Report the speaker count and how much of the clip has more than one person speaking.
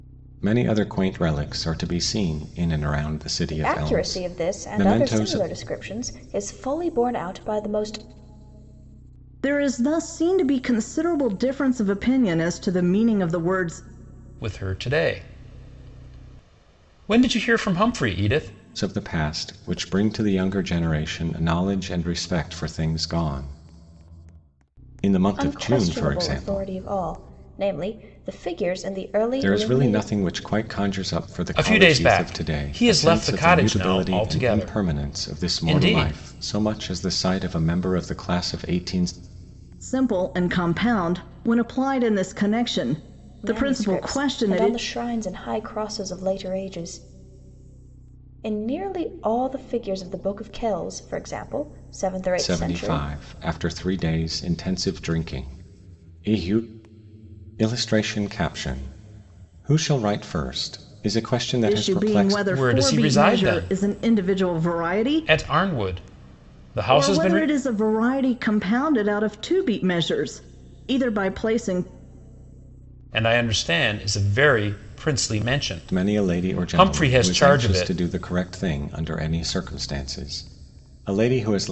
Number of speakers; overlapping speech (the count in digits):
4, about 21%